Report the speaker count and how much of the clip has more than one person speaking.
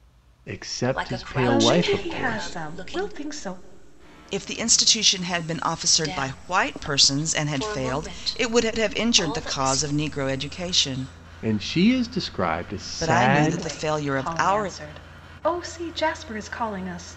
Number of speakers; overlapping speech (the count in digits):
4, about 40%